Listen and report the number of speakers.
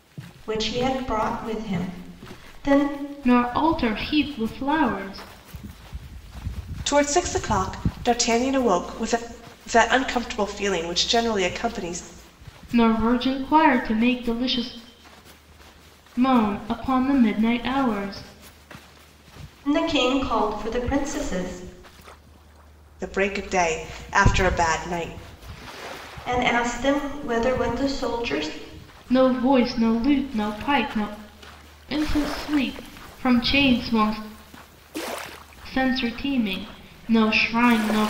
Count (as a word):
three